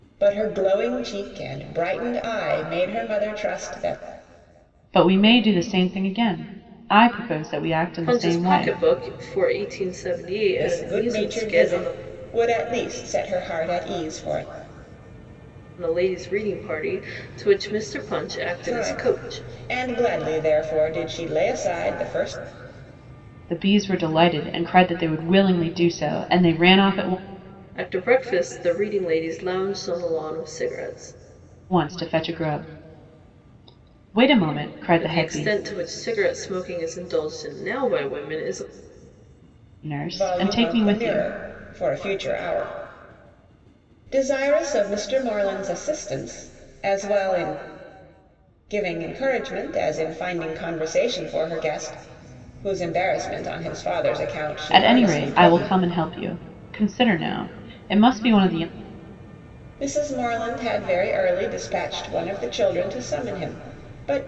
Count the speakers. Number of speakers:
3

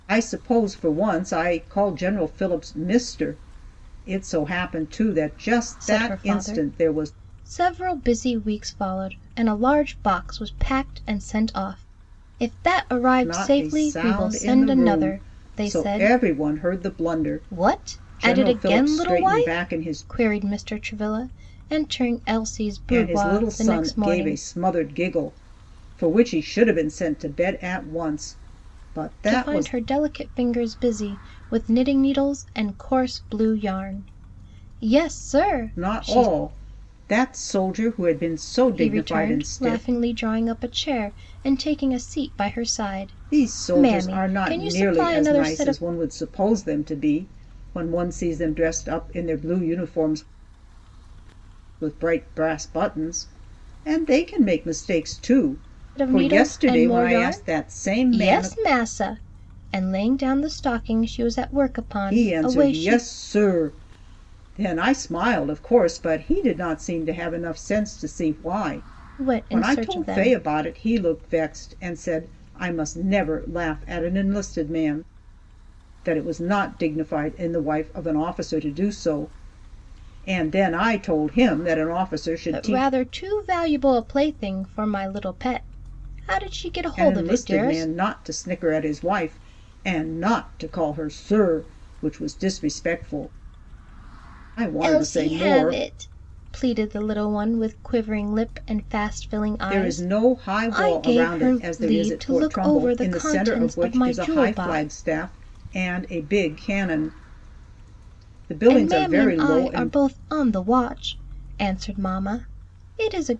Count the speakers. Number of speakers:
2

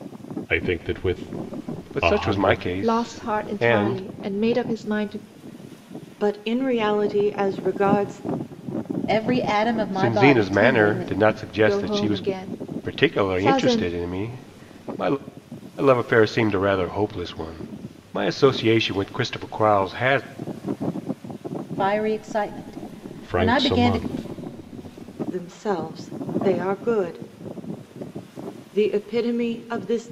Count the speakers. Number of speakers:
5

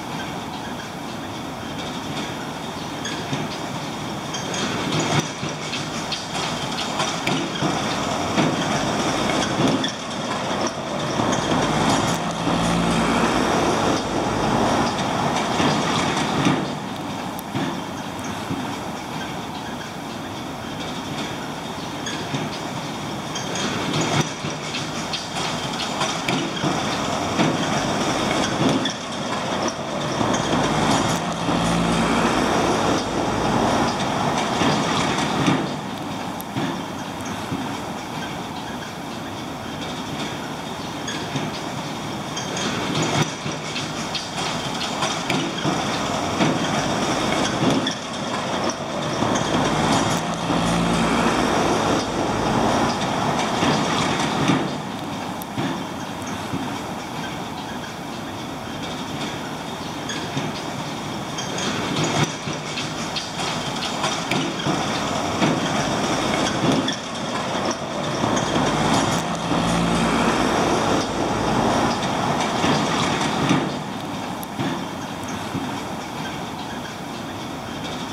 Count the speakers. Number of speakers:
0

